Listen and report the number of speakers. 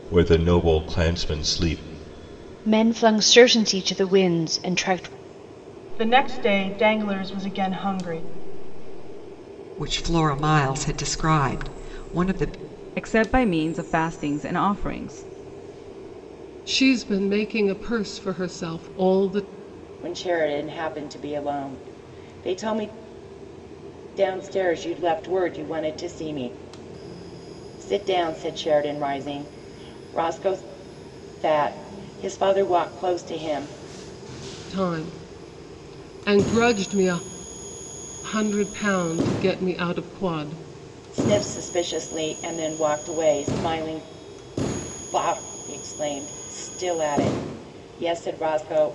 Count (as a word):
seven